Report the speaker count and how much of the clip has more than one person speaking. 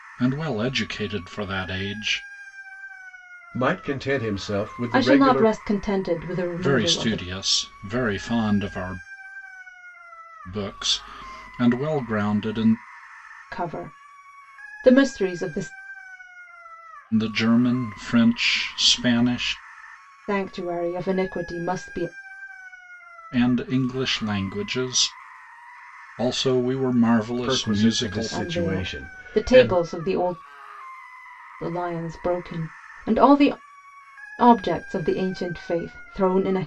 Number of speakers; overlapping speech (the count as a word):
three, about 10%